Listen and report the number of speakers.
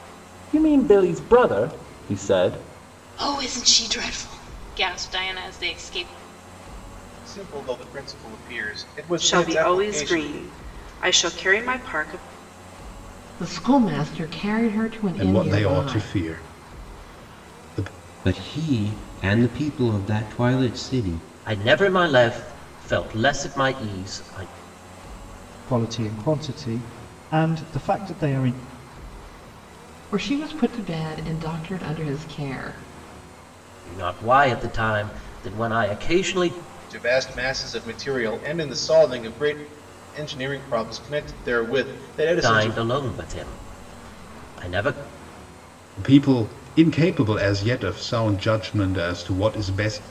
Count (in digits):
9